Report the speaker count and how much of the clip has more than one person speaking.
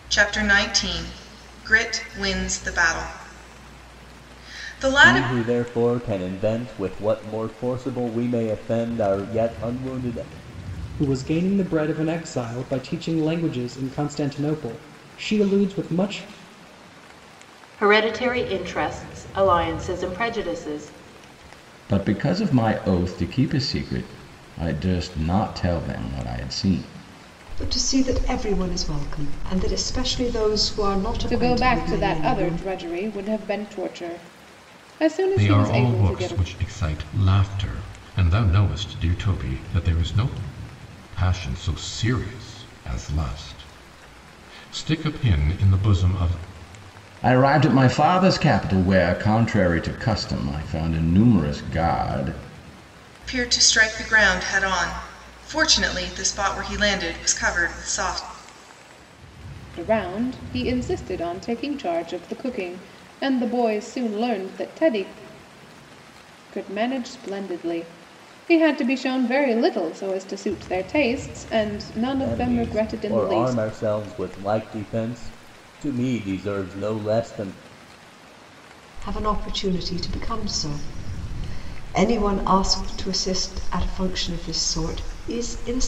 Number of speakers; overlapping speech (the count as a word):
eight, about 5%